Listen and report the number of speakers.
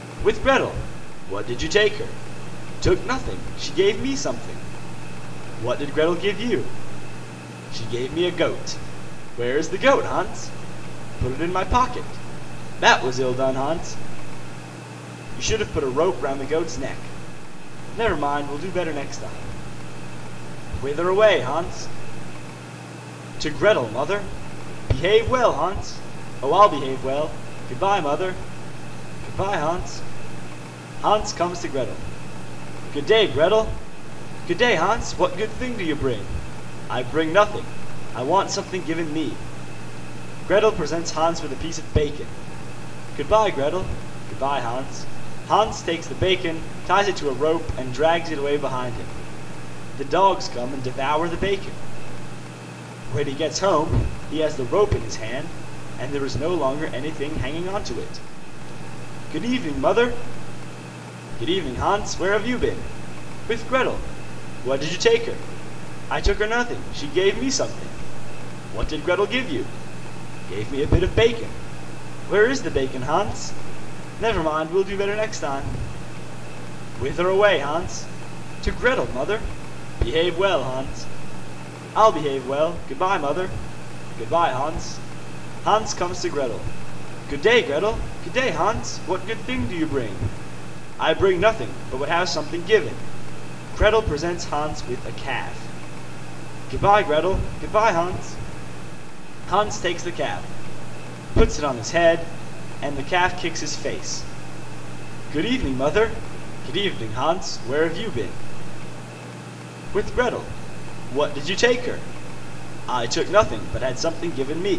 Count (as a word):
one